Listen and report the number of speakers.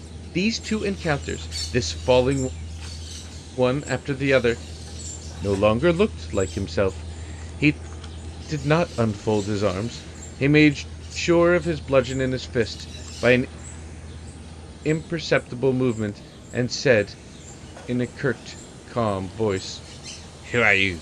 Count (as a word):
one